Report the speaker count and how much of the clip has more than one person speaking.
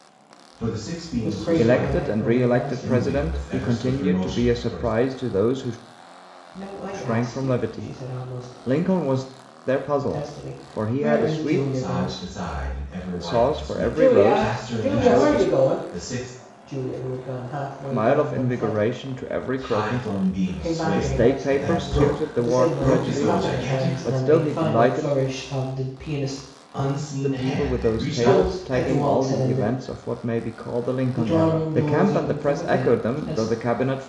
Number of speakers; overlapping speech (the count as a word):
three, about 63%